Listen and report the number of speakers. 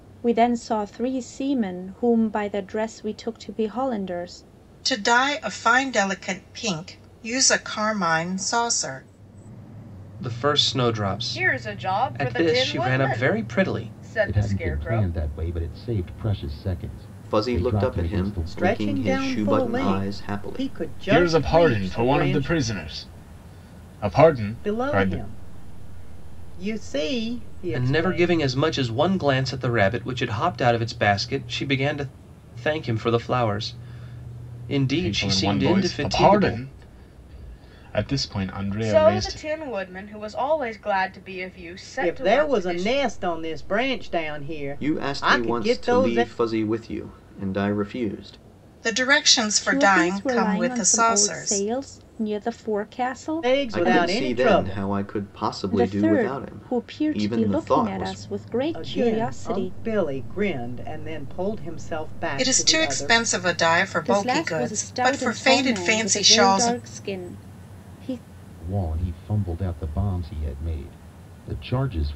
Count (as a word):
eight